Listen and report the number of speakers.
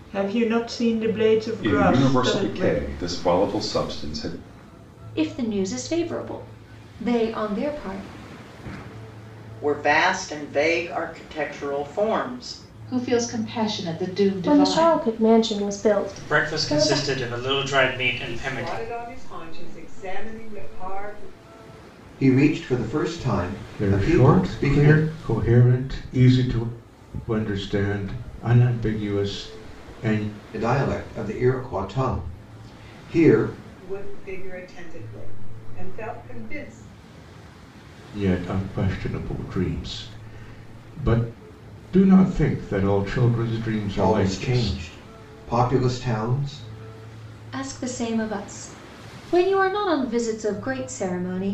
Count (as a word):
ten